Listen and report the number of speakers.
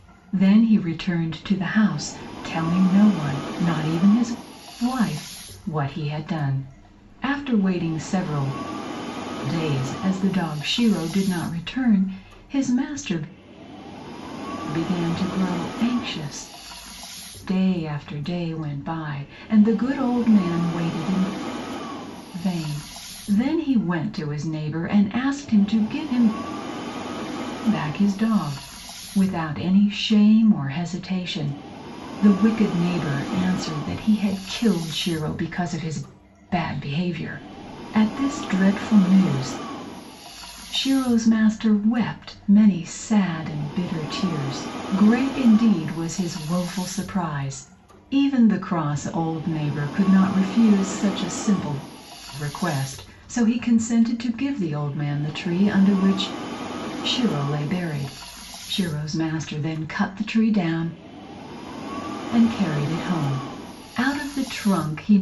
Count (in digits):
1